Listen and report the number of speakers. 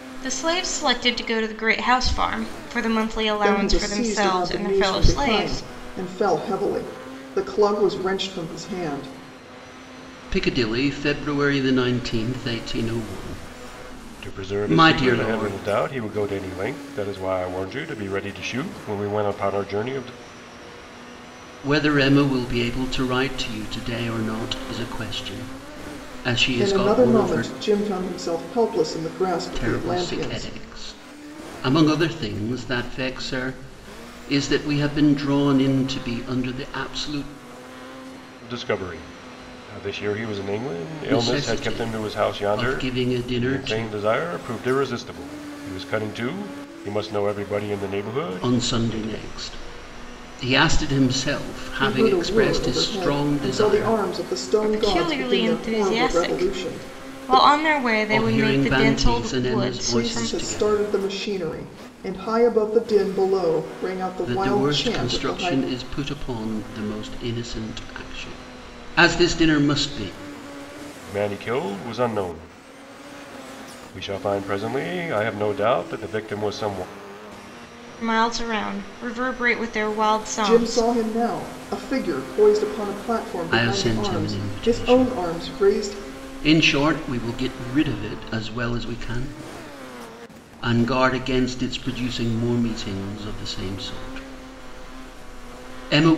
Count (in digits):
4